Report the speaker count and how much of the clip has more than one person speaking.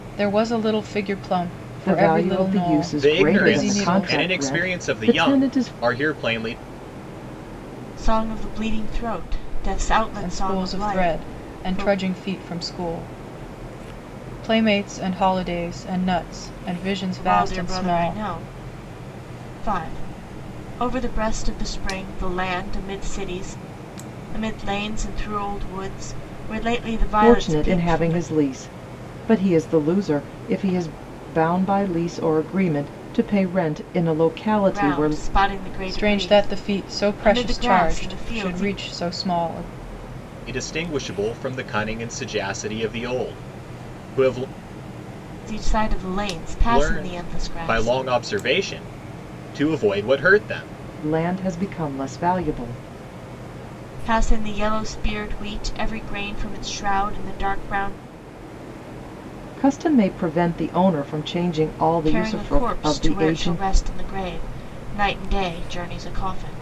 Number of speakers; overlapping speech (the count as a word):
four, about 22%